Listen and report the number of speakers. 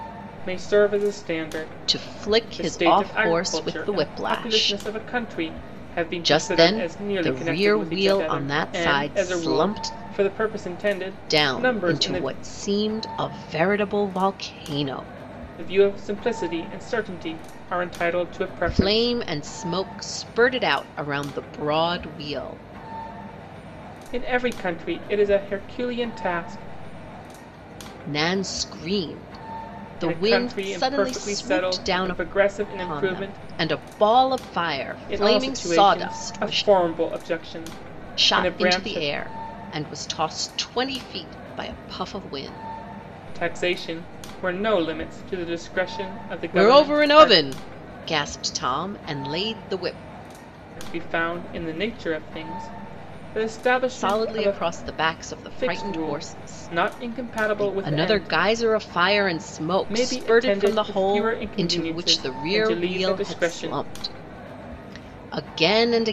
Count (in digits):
2